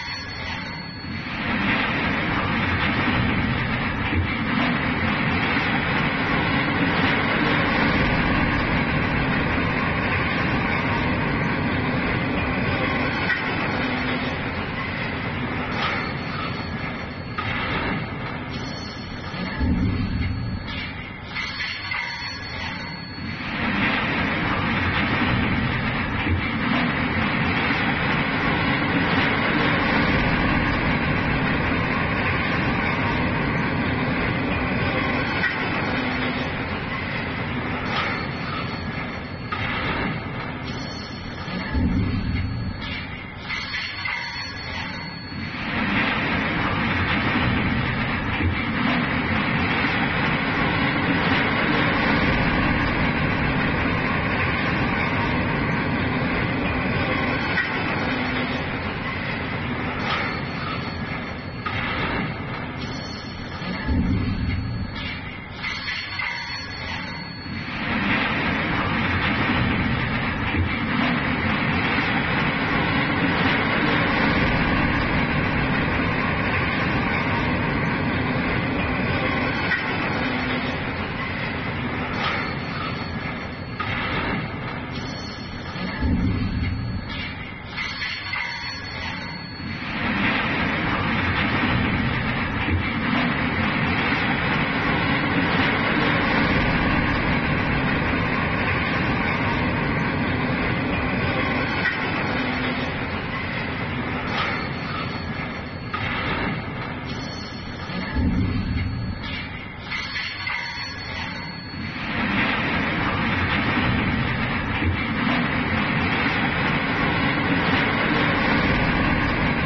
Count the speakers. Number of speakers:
zero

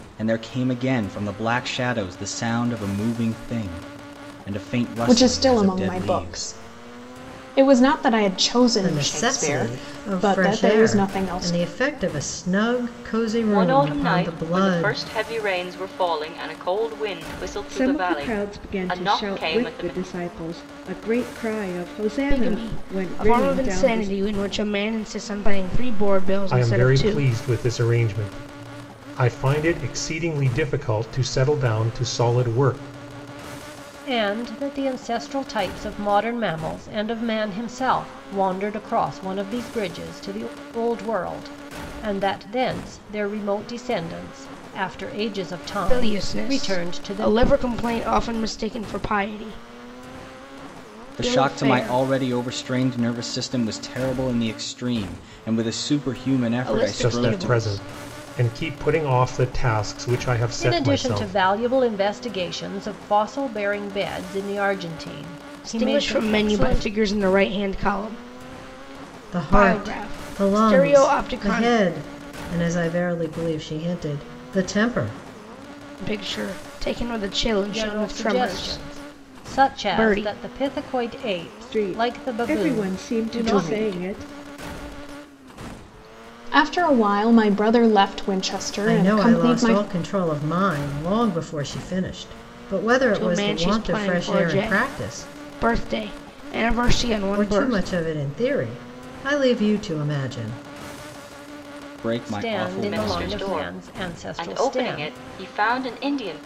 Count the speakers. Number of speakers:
eight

